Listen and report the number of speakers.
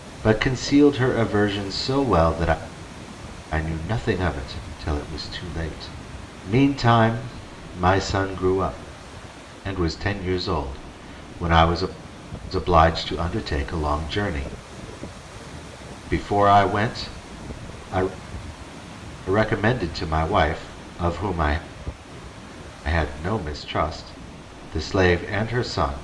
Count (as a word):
one